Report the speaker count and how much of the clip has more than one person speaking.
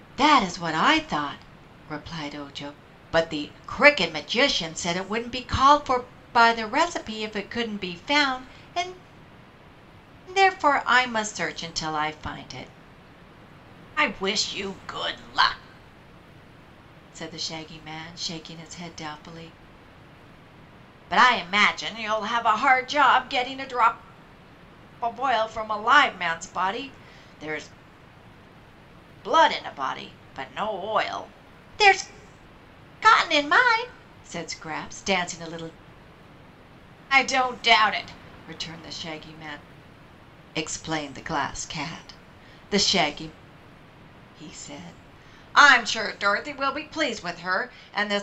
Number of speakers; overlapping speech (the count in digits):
1, no overlap